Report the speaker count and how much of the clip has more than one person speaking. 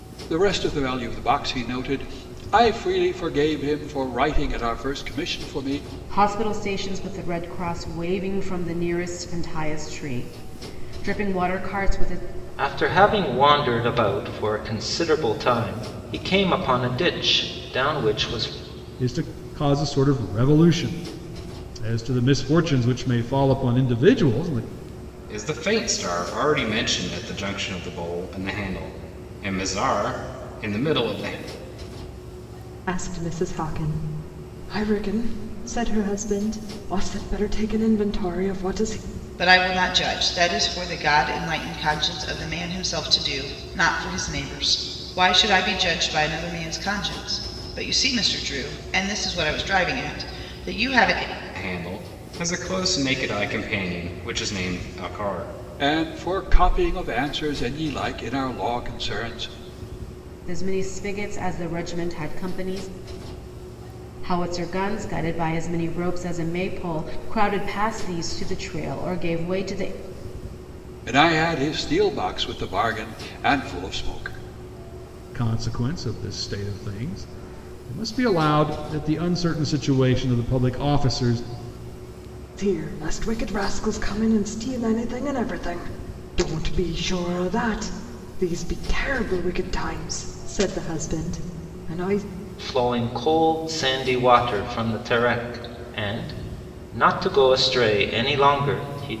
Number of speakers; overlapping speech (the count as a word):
seven, no overlap